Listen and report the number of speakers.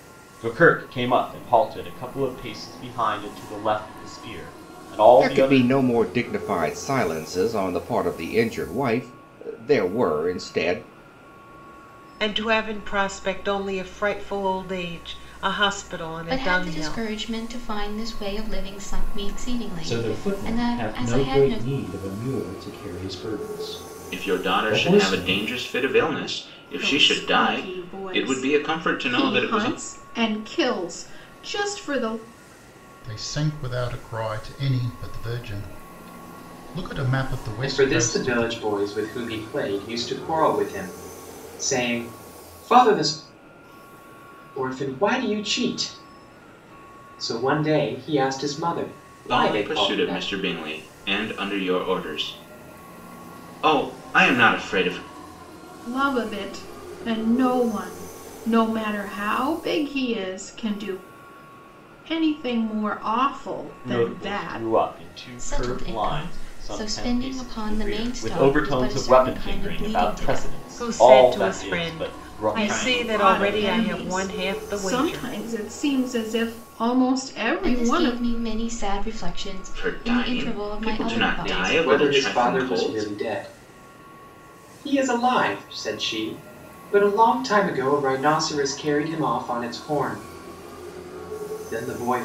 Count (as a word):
nine